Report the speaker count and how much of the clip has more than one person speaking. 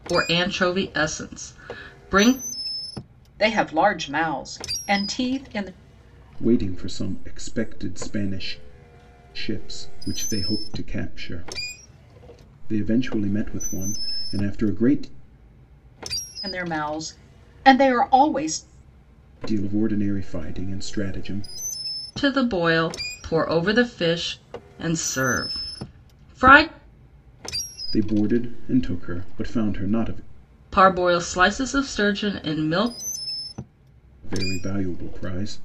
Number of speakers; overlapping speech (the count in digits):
3, no overlap